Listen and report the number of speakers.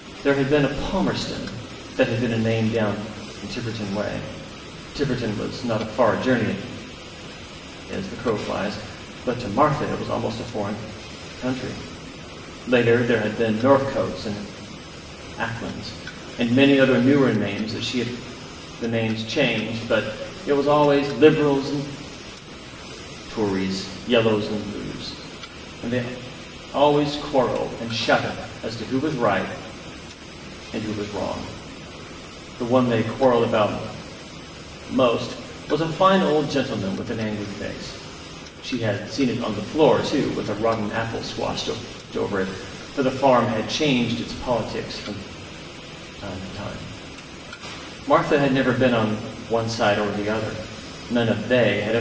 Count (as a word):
one